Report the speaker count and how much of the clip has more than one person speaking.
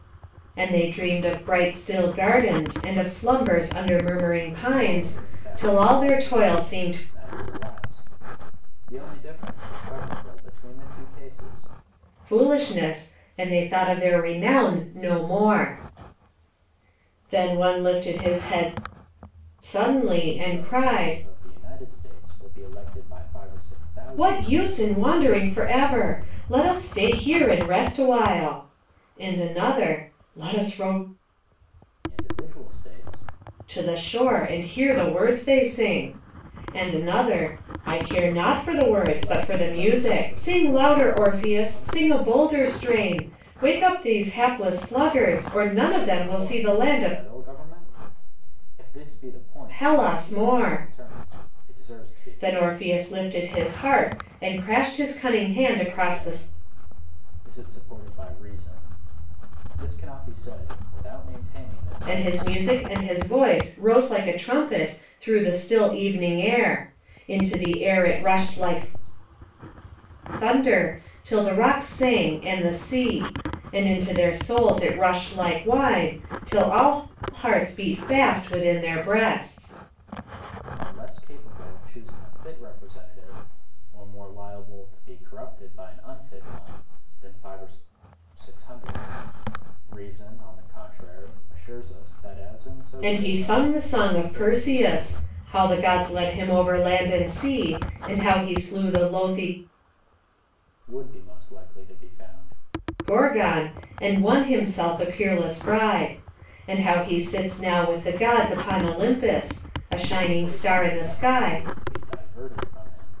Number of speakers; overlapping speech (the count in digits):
2, about 17%